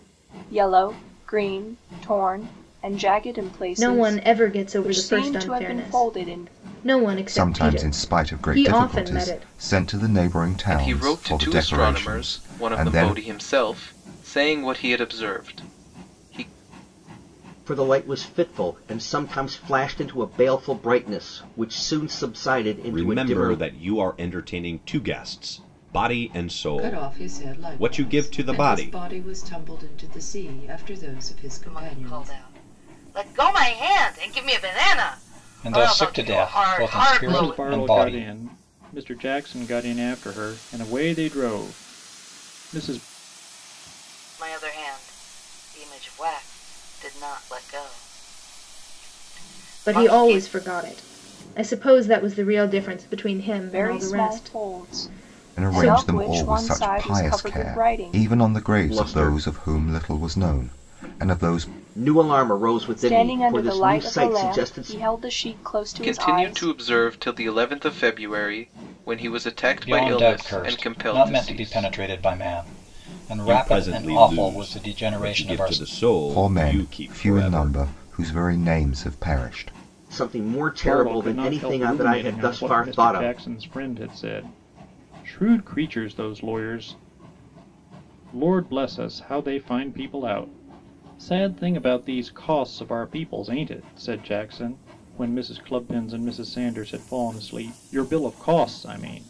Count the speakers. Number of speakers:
10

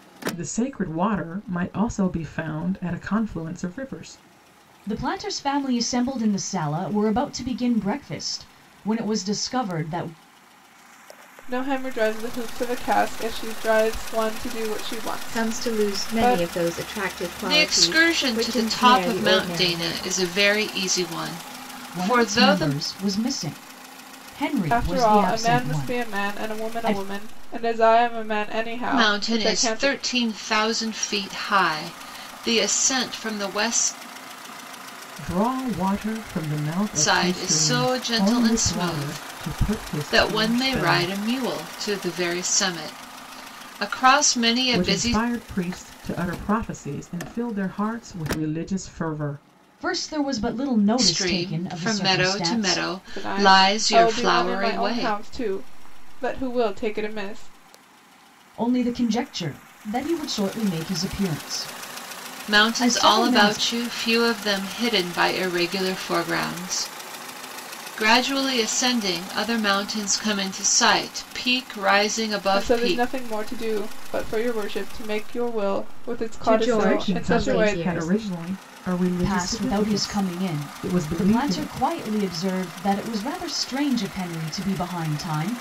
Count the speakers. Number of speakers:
5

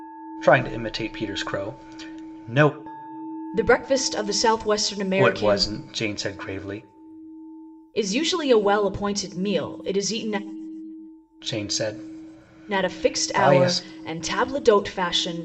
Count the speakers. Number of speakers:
2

